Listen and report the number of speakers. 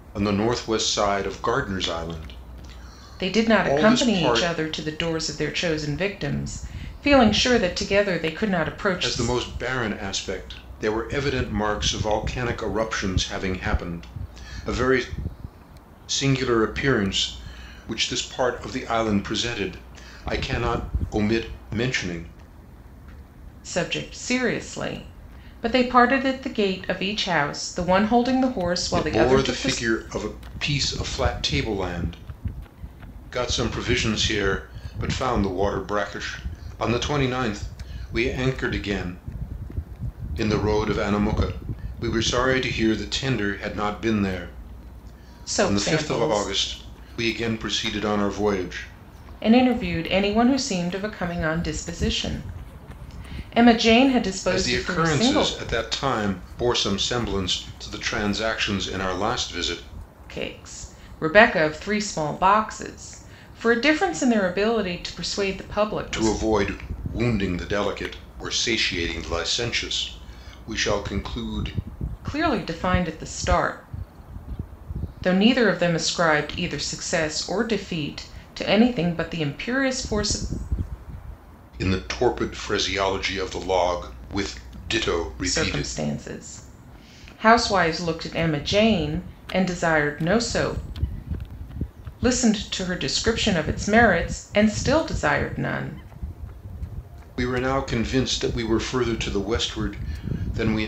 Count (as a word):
two